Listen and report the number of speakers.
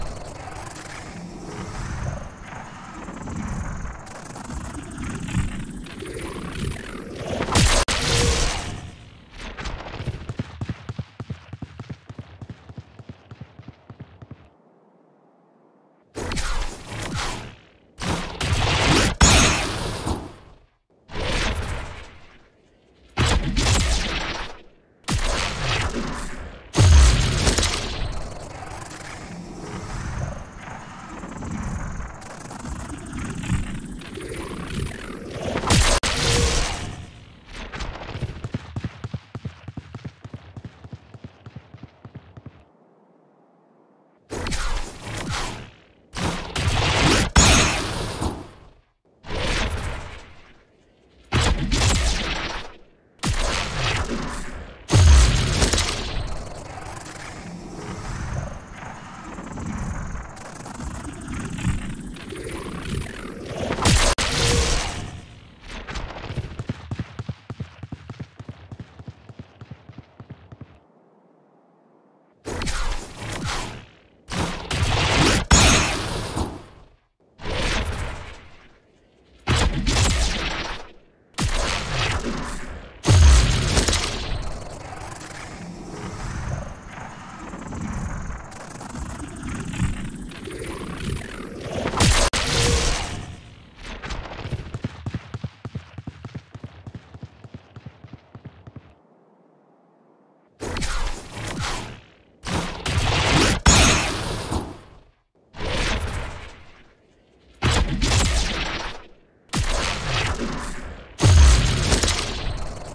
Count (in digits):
0